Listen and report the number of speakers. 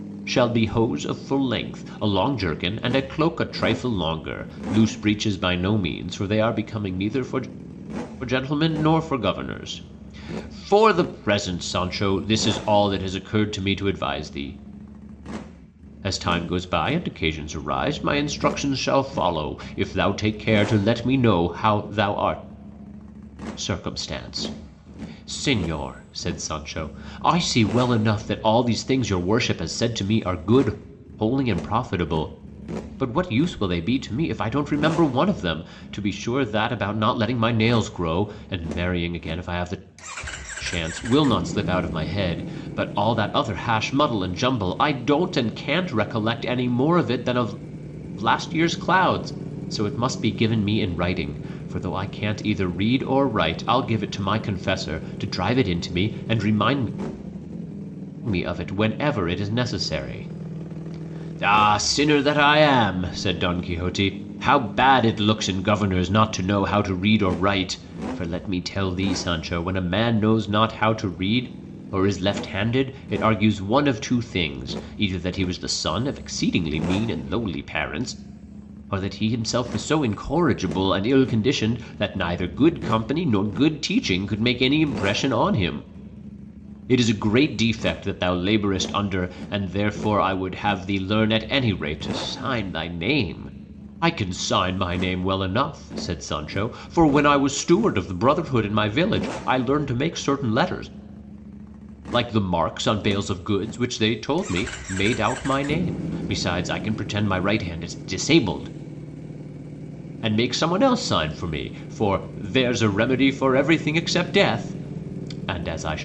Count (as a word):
one